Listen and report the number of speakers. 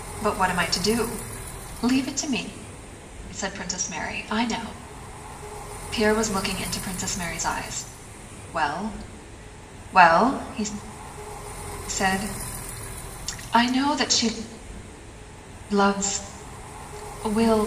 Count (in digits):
1